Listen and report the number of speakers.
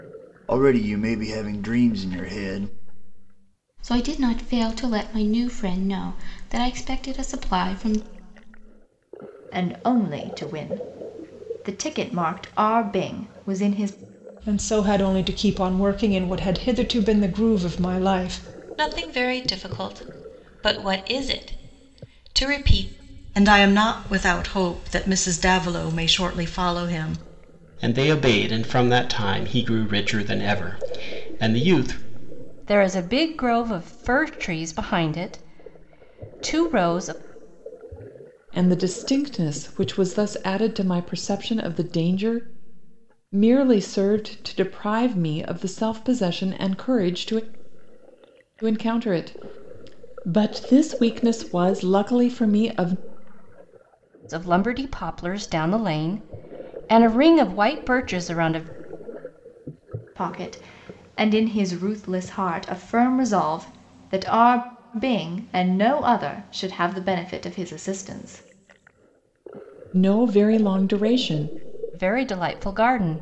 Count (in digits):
9